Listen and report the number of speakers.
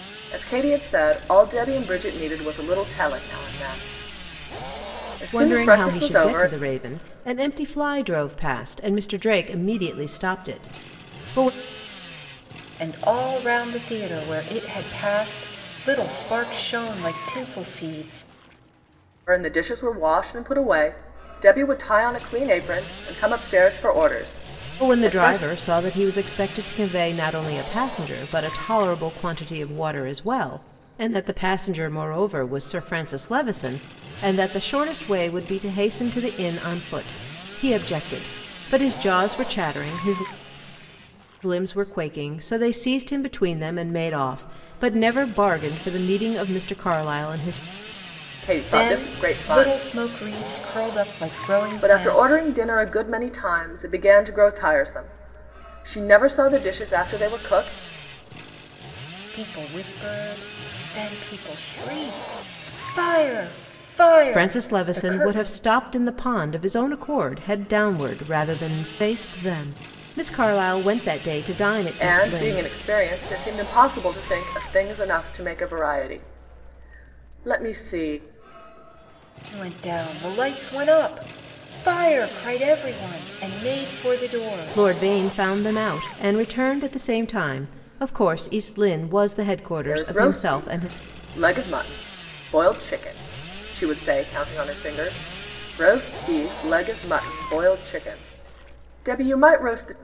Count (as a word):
three